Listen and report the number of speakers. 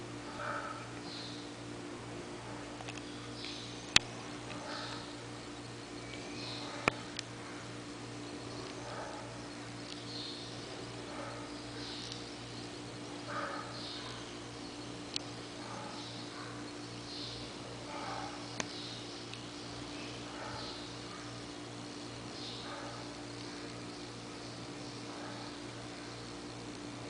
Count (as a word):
zero